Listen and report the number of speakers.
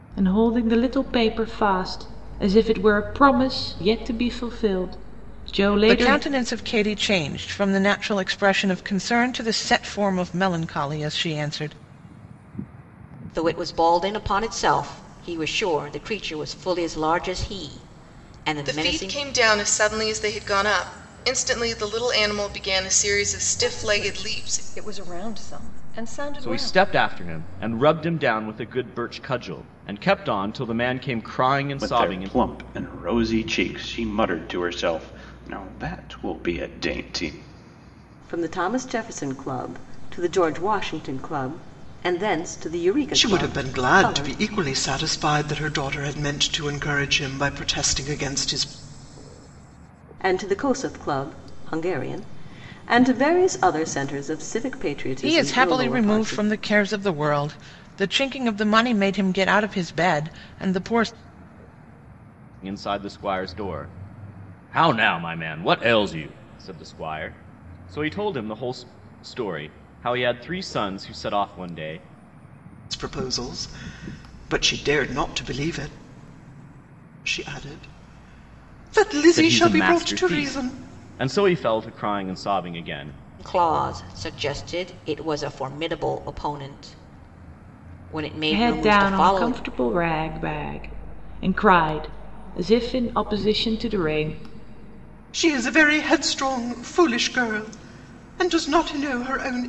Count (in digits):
9